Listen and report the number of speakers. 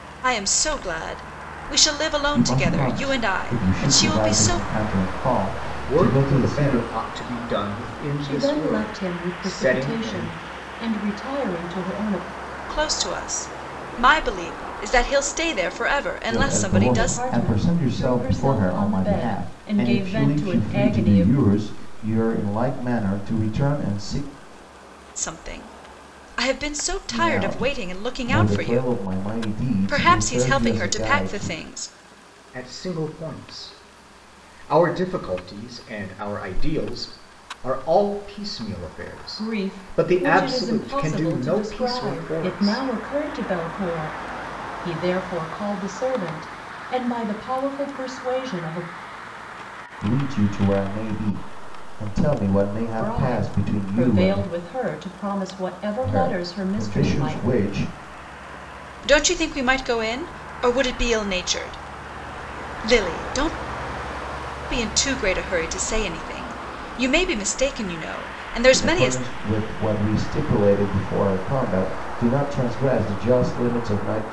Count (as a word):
four